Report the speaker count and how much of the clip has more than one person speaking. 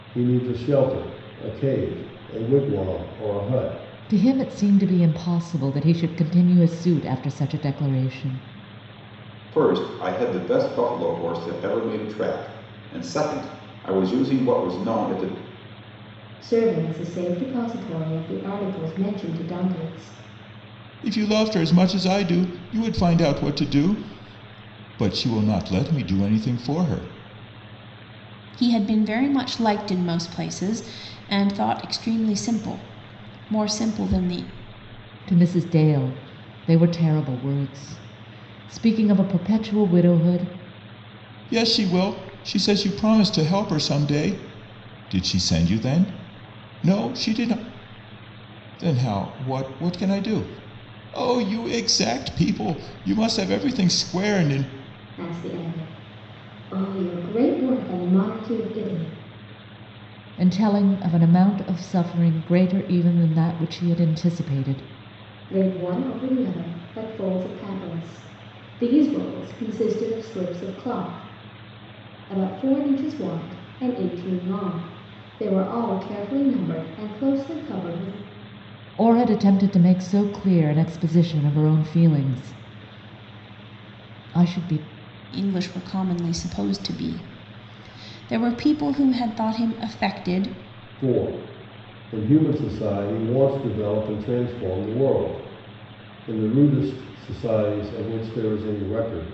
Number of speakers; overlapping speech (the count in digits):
6, no overlap